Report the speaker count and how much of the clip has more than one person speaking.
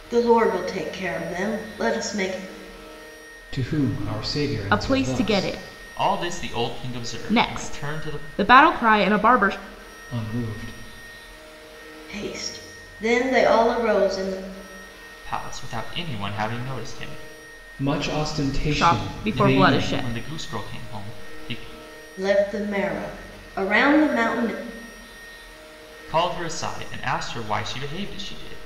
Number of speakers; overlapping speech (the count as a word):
four, about 12%